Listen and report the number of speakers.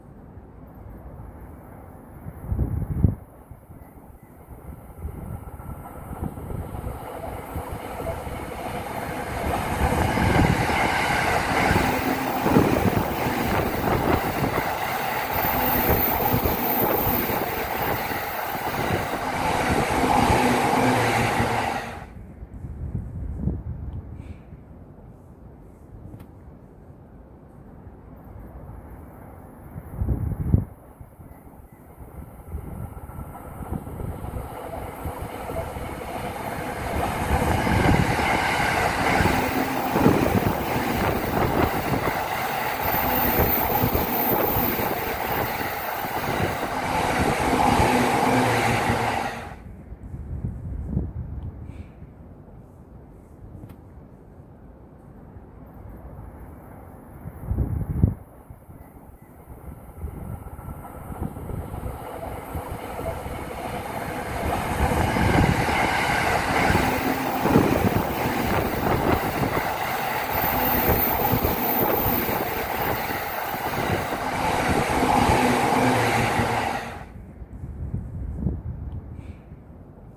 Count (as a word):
zero